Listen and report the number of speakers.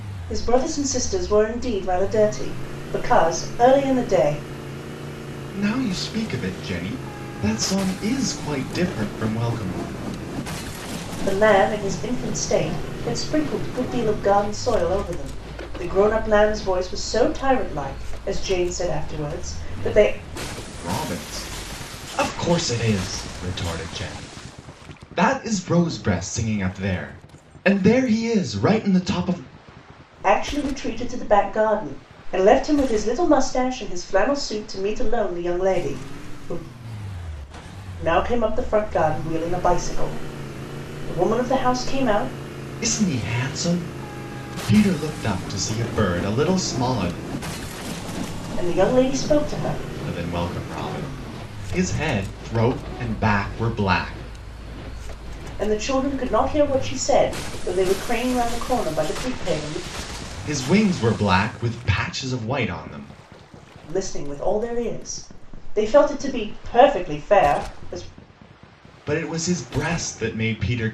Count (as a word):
two